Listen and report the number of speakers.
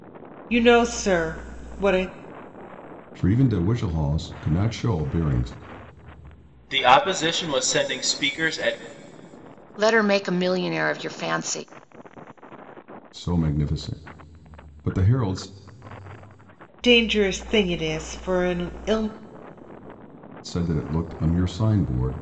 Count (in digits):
4